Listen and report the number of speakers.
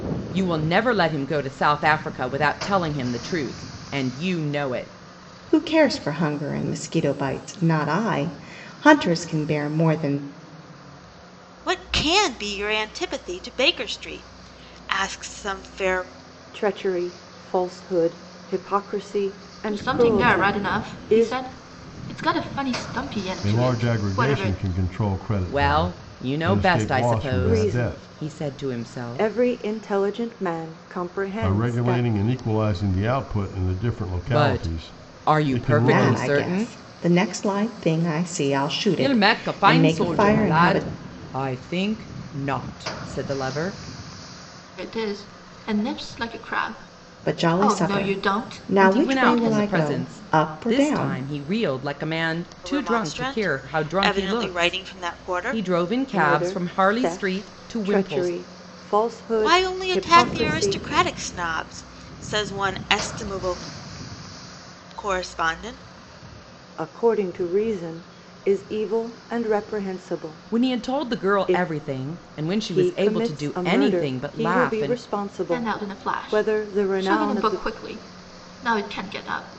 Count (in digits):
6